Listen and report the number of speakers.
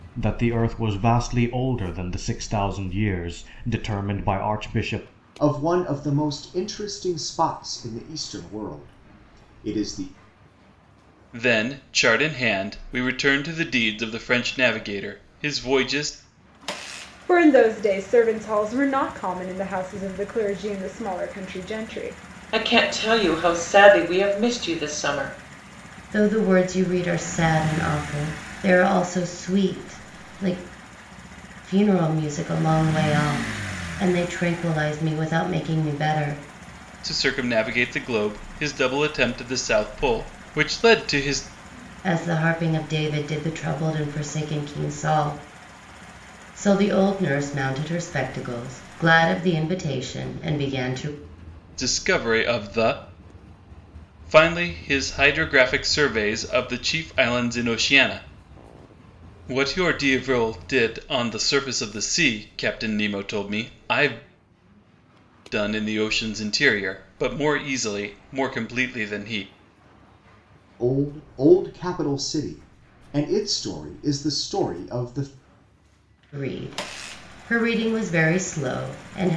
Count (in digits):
6